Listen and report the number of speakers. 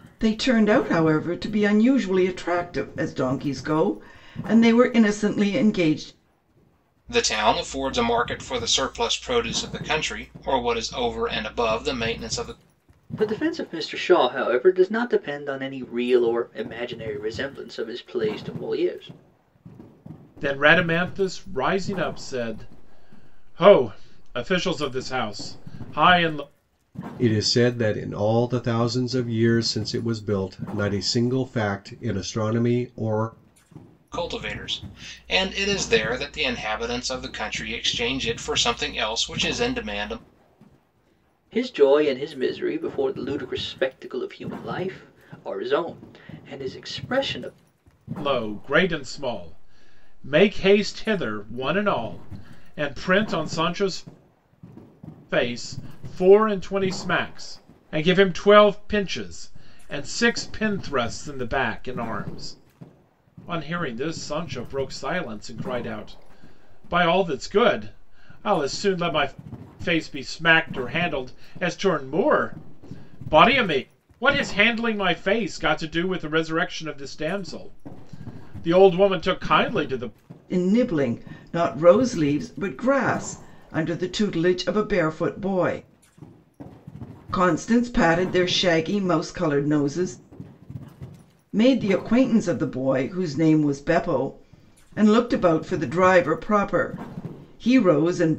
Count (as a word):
five